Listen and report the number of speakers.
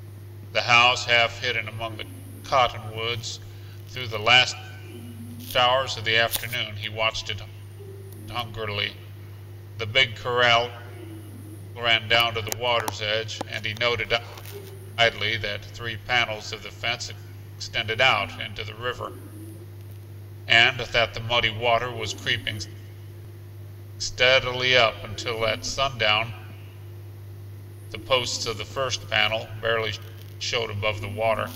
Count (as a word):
one